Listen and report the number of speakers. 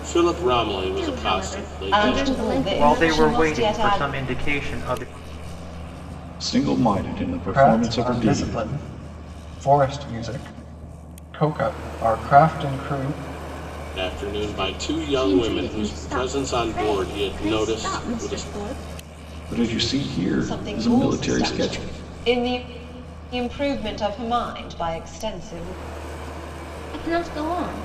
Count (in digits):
6